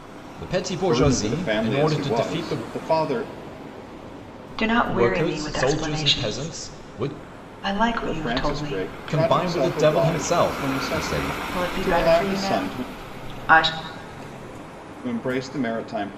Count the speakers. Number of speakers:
three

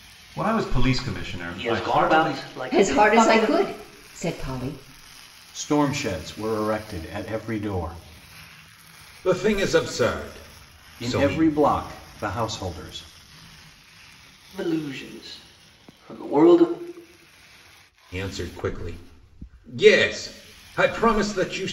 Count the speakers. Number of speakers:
five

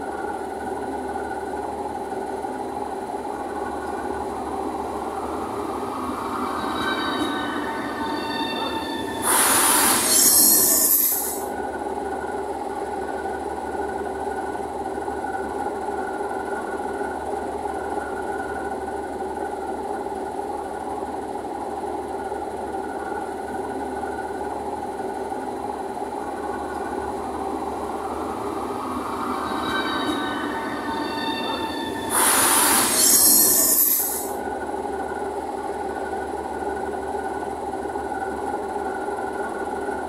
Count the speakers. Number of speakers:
zero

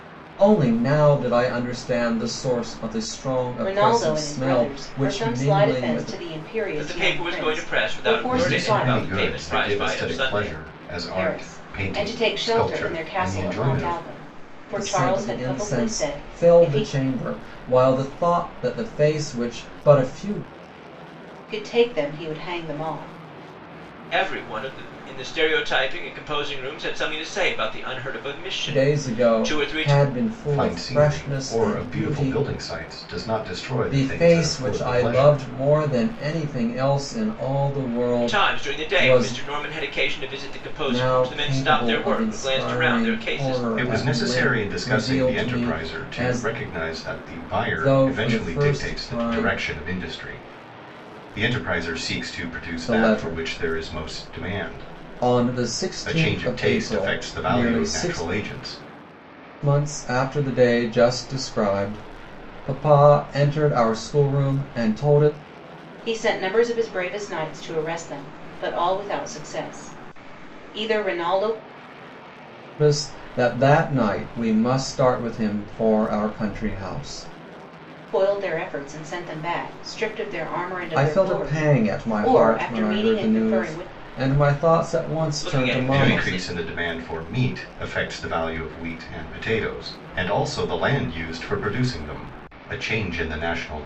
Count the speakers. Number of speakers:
four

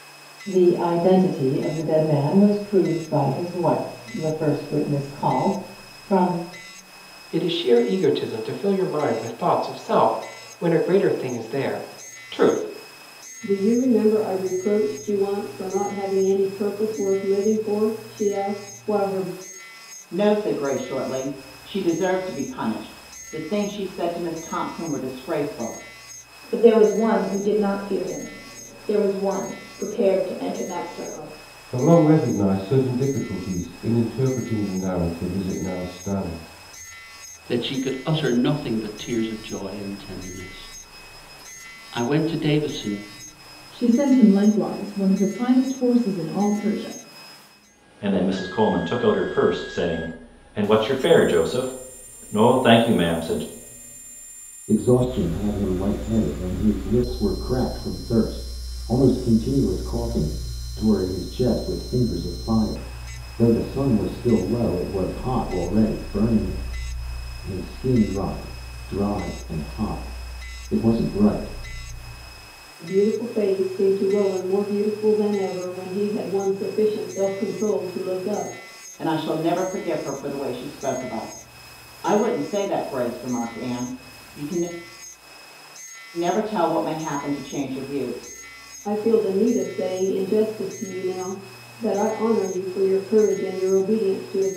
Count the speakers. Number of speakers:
ten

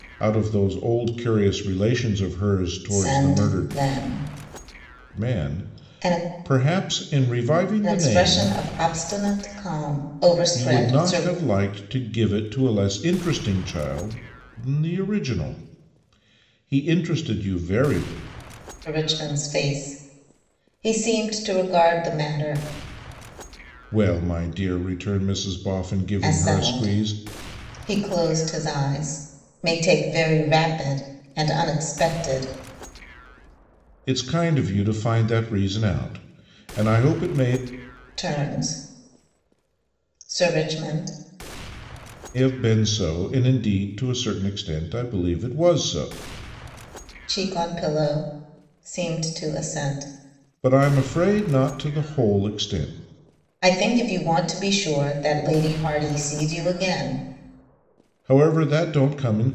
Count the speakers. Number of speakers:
two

